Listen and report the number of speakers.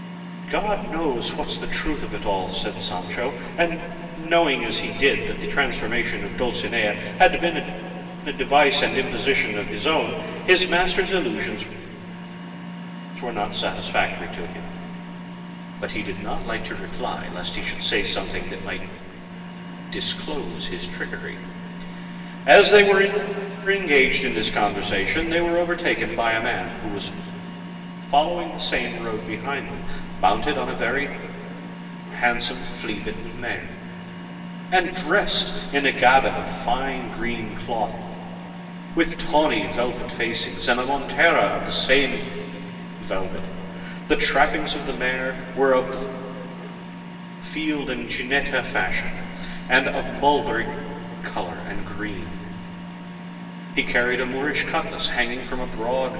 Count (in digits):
1